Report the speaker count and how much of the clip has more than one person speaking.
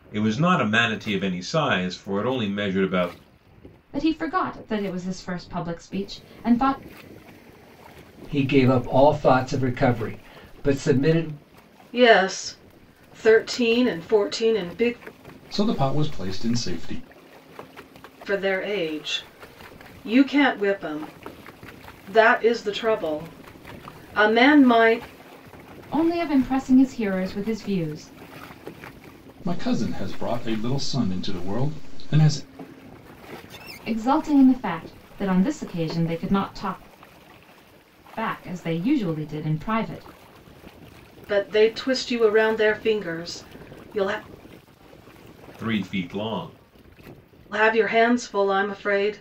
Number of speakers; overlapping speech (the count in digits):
5, no overlap